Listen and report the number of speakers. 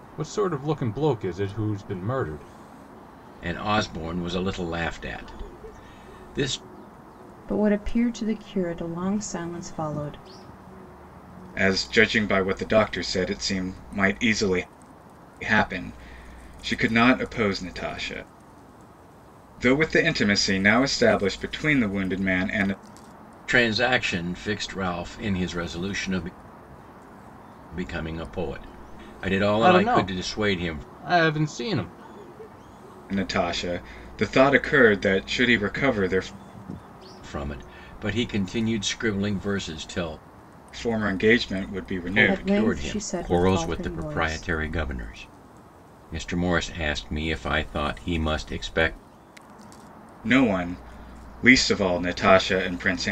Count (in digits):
4